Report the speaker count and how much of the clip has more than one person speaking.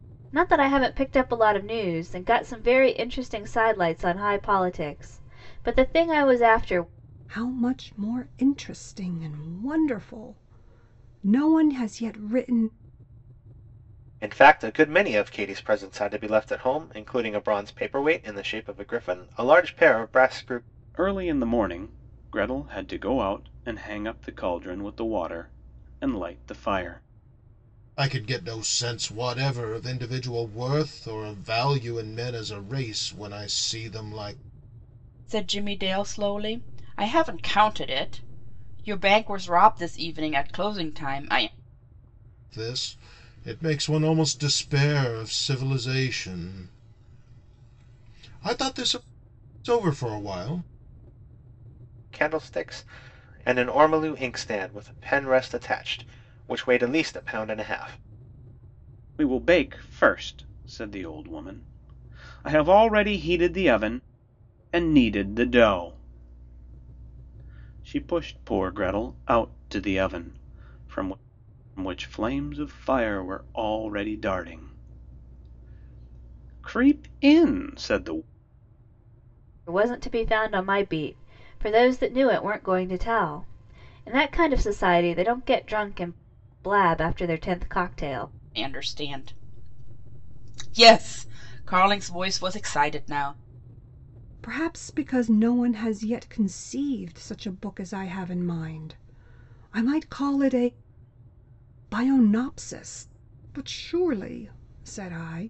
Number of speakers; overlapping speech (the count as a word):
six, no overlap